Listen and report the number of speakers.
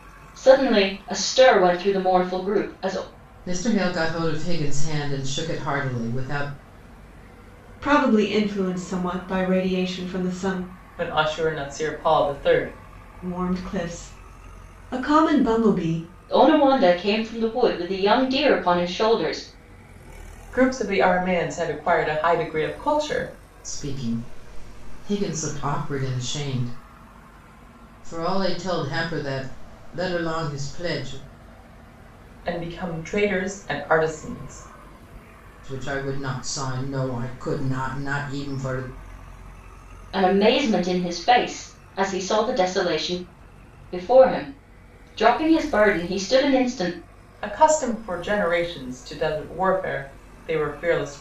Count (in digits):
4